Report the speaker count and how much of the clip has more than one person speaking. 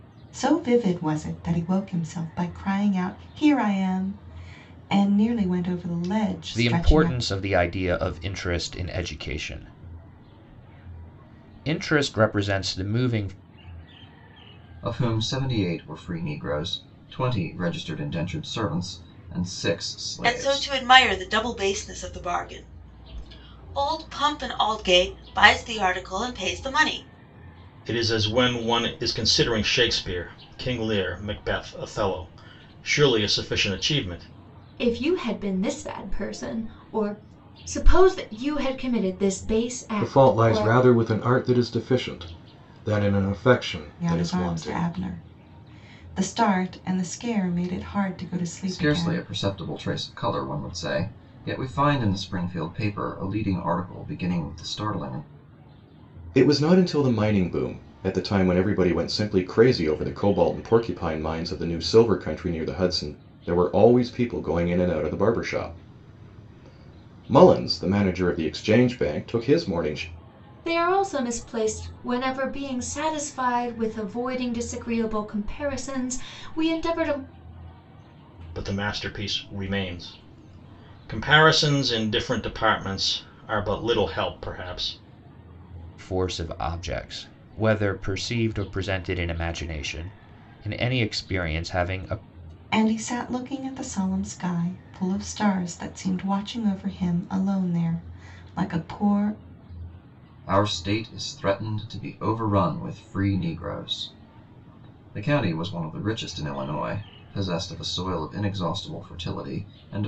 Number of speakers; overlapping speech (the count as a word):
seven, about 3%